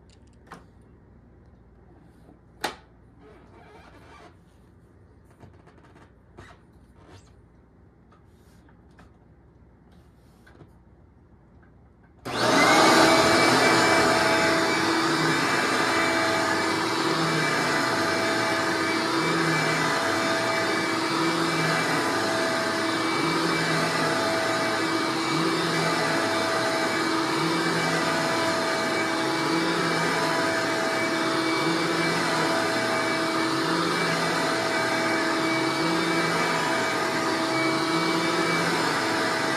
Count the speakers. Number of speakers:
0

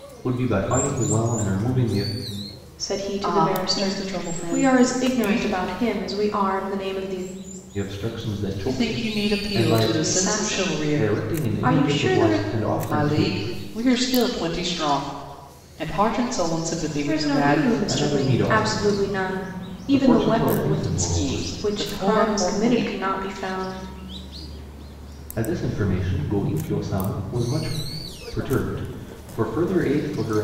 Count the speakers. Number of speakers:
3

